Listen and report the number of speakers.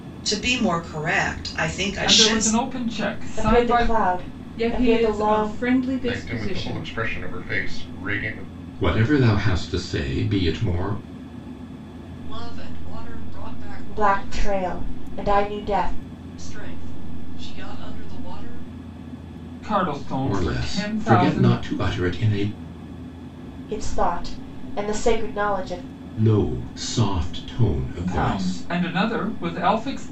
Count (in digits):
7